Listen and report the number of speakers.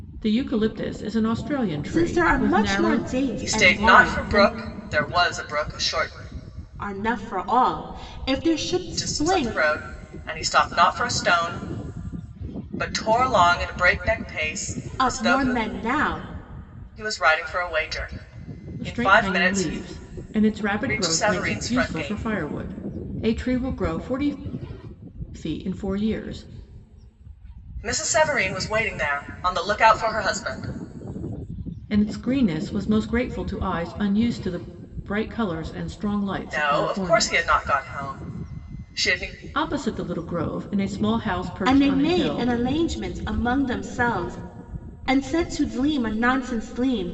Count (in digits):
3